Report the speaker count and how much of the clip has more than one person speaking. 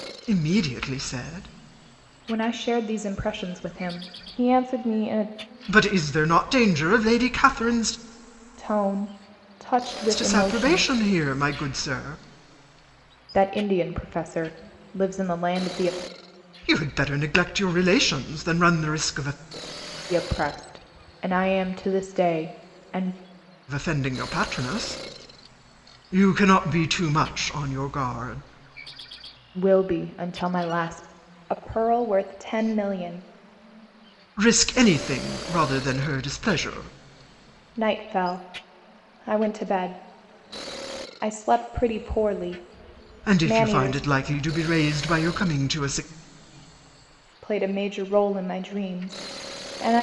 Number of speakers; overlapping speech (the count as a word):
two, about 3%